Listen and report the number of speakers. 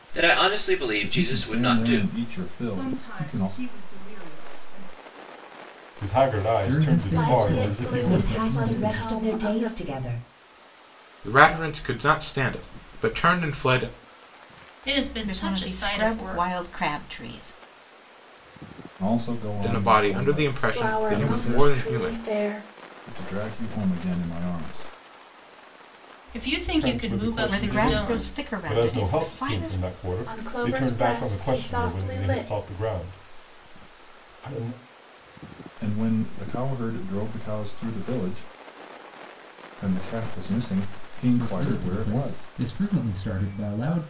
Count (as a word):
ten